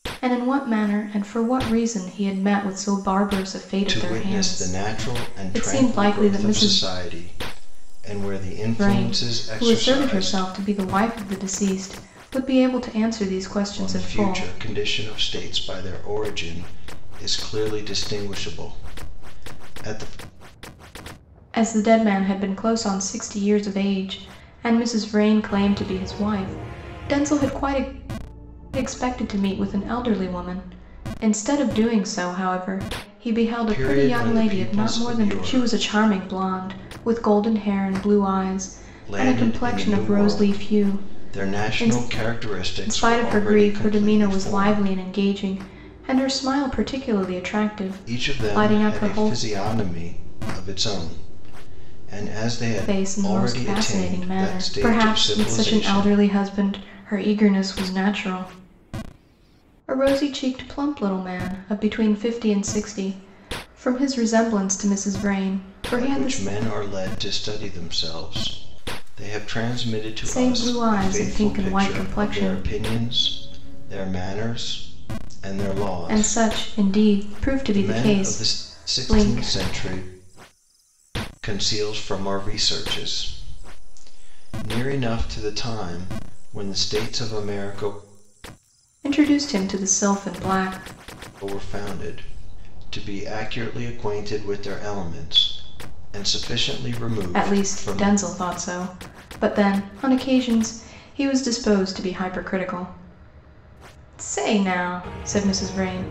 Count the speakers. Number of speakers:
2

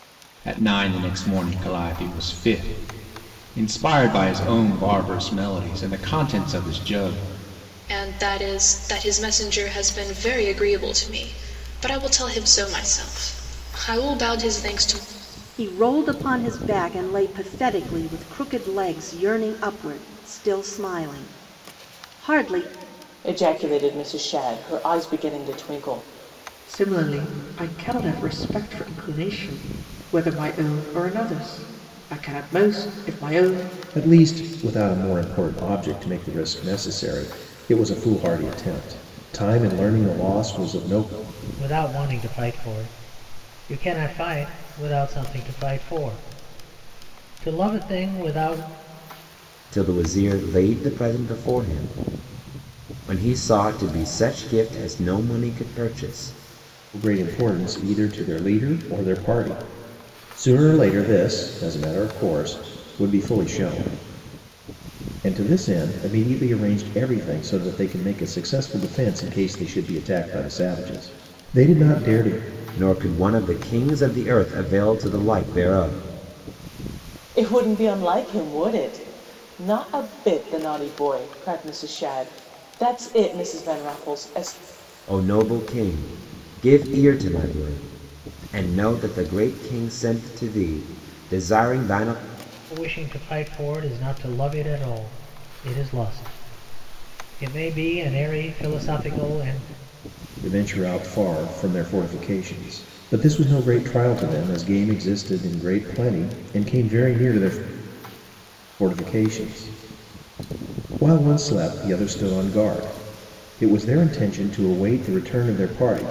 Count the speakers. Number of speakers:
8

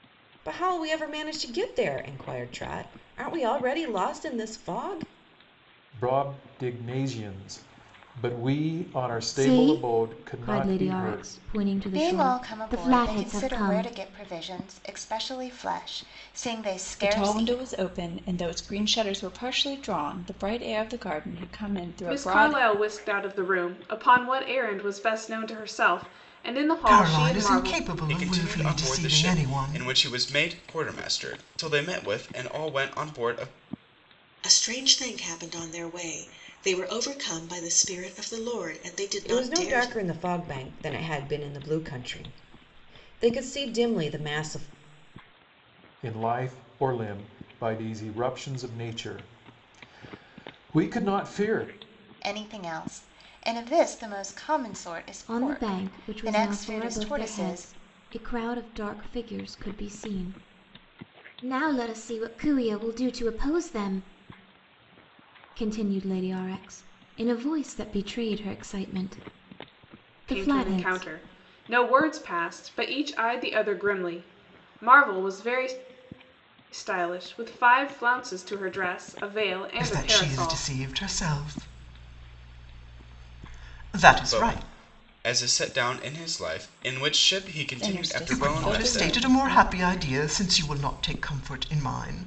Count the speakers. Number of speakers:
9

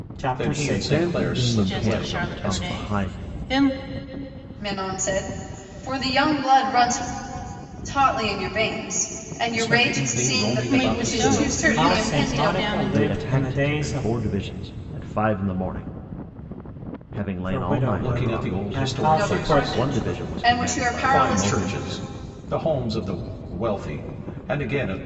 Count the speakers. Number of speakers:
5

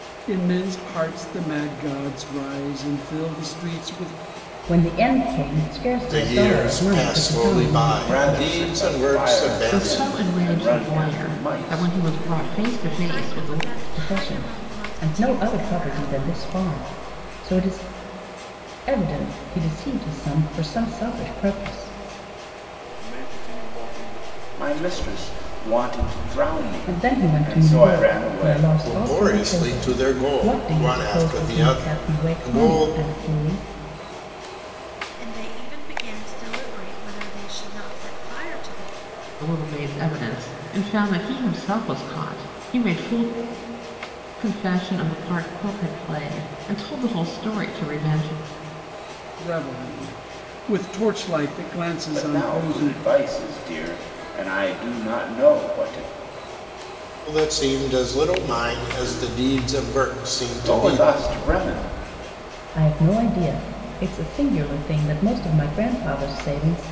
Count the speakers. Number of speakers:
7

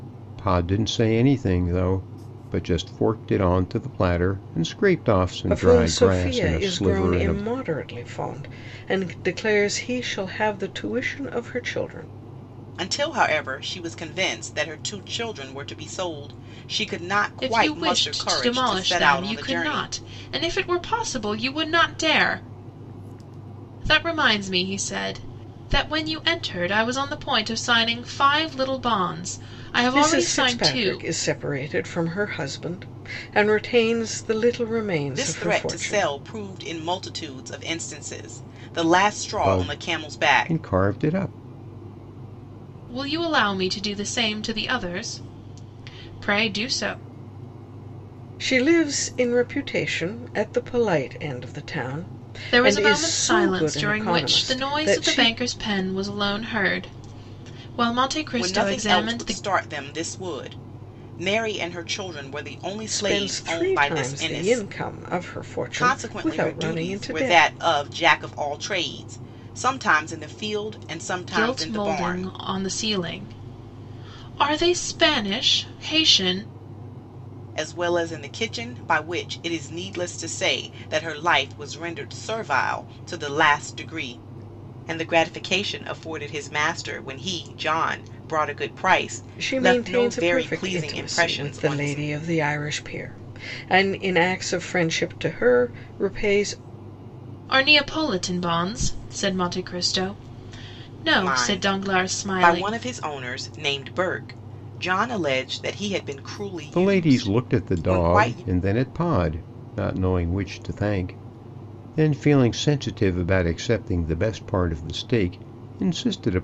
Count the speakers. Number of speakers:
4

